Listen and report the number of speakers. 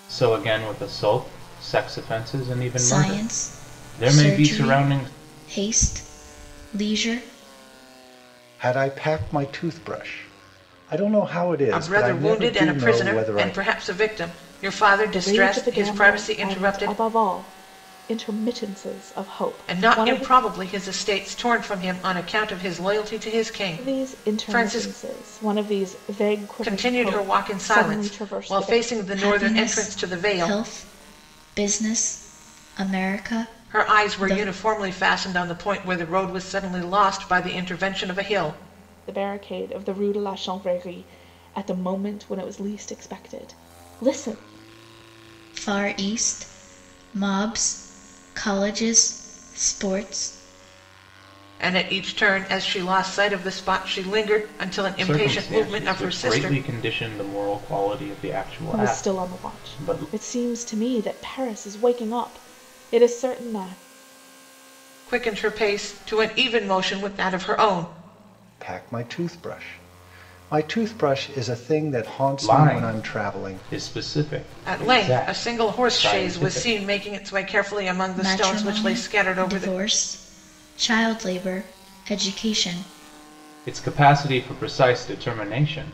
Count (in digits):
5